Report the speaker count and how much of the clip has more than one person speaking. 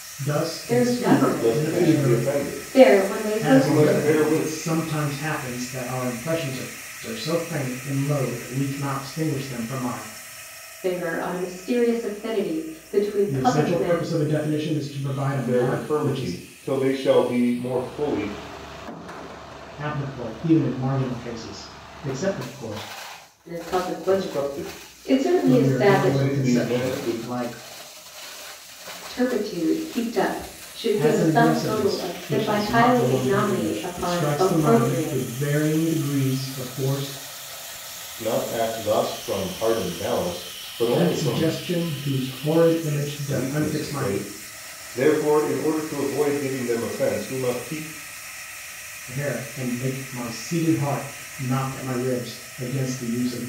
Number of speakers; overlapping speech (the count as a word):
three, about 28%